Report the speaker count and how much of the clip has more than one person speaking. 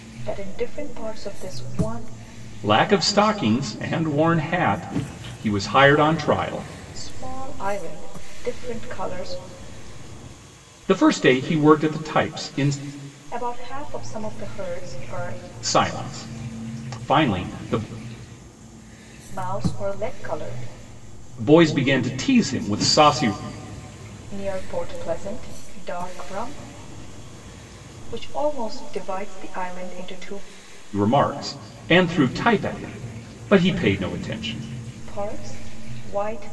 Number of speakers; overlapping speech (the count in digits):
2, no overlap